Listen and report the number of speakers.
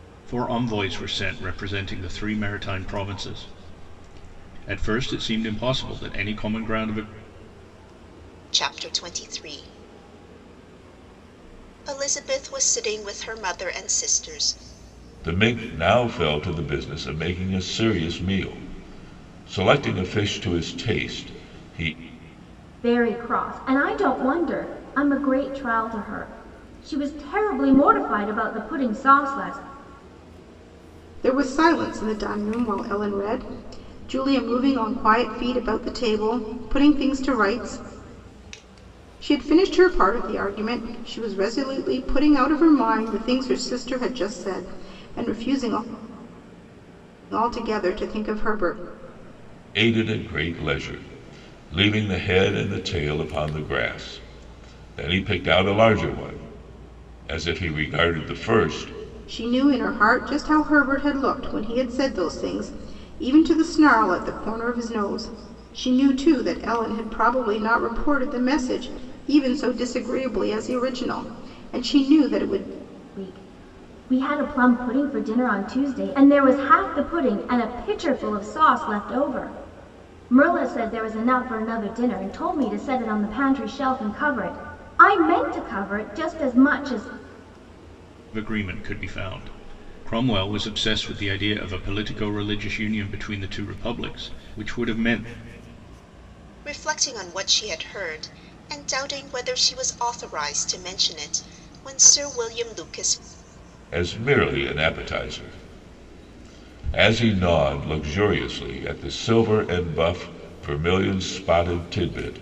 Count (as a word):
five